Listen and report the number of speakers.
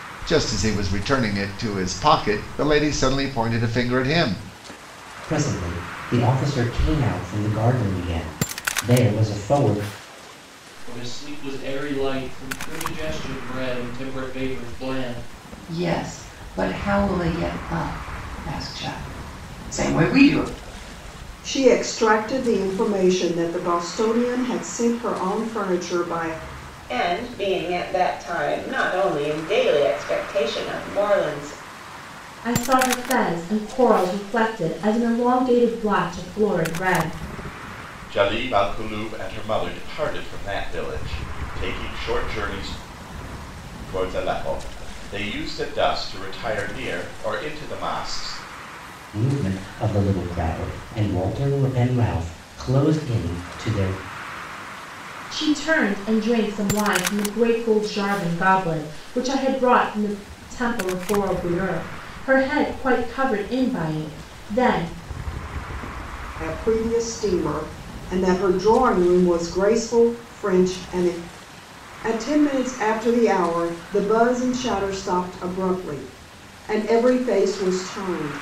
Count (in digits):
8